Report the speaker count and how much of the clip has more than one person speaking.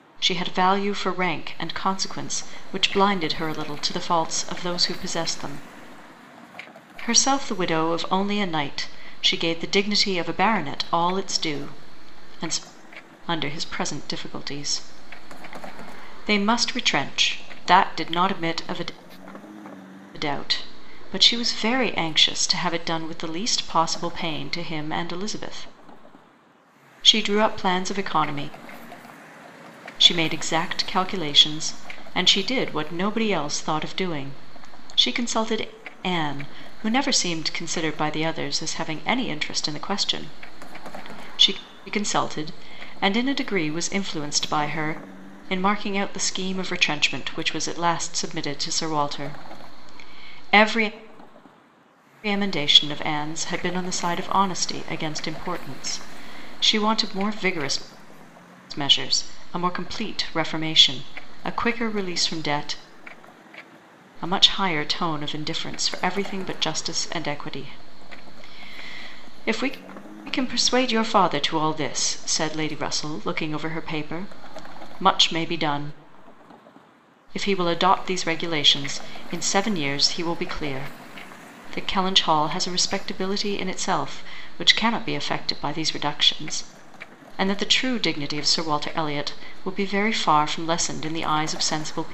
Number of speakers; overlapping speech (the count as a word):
one, no overlap